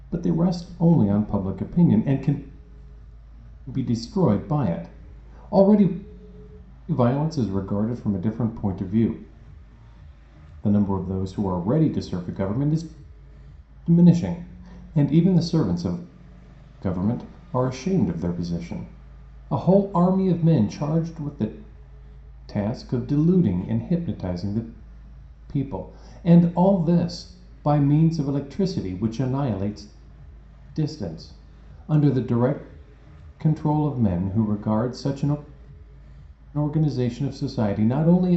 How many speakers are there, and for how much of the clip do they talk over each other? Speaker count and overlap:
1, no overlap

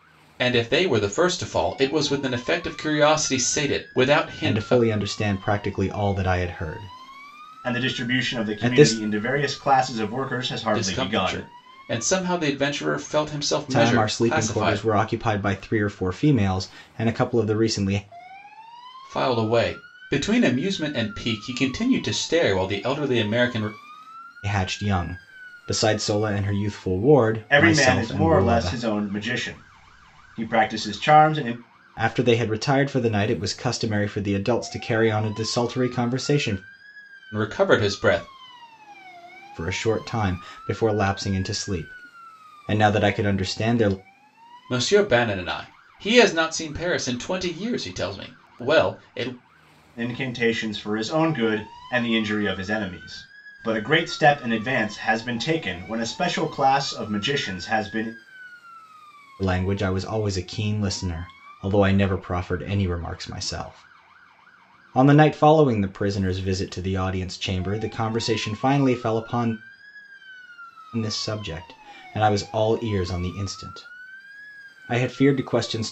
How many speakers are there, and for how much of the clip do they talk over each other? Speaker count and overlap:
3, about 7%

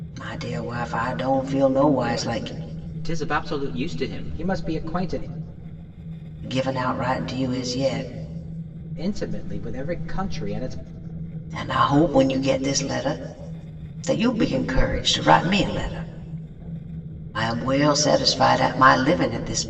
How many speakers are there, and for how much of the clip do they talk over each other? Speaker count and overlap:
2, no overlap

